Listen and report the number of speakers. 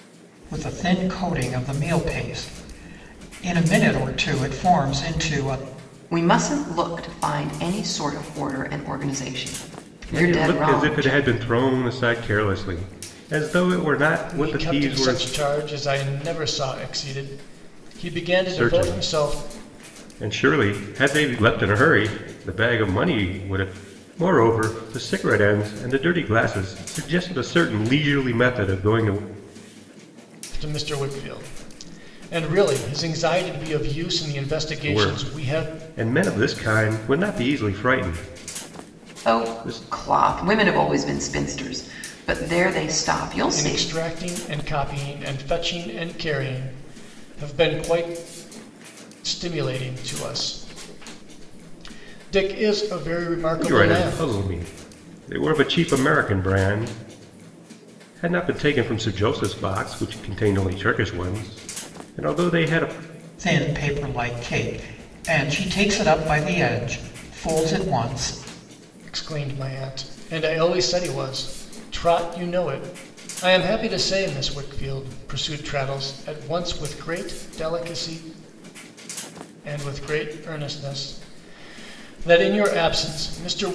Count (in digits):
4